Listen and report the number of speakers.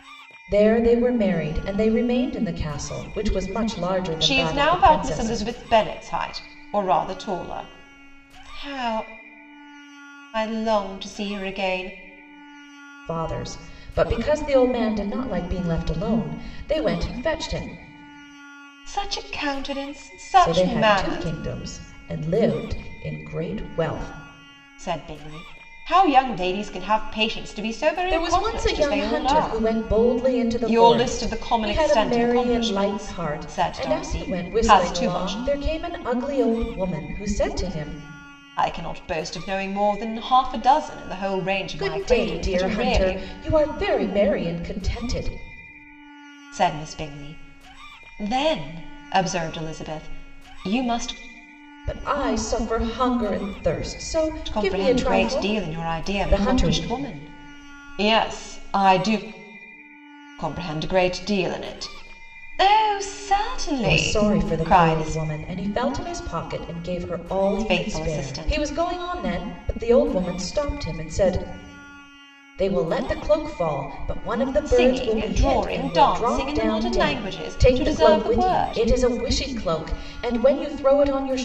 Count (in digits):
2